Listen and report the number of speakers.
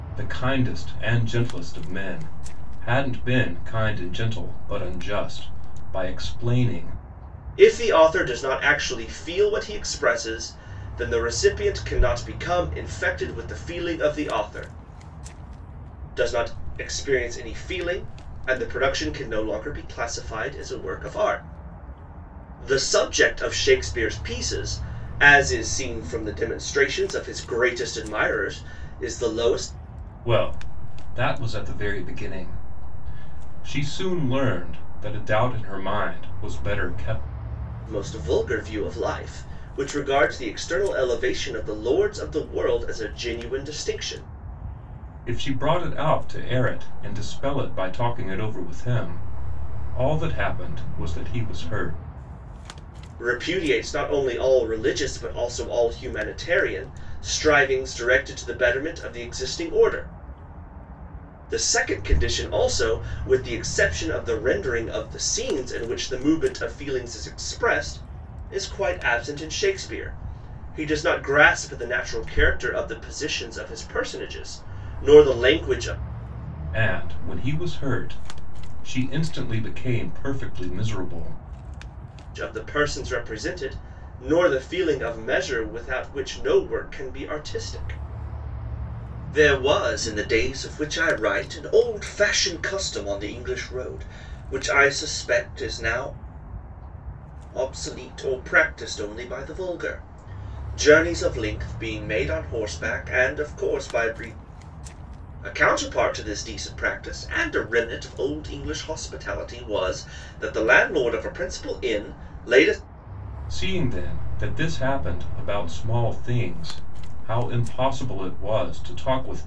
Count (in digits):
2